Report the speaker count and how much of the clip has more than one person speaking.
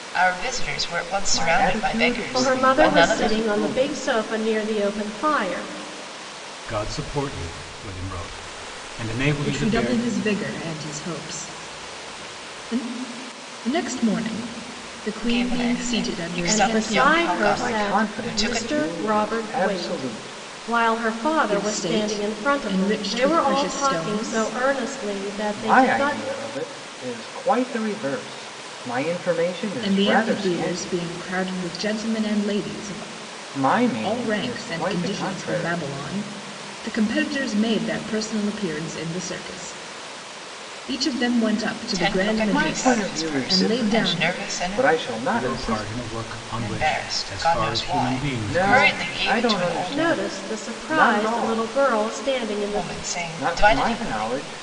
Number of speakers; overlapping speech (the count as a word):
five, about 48%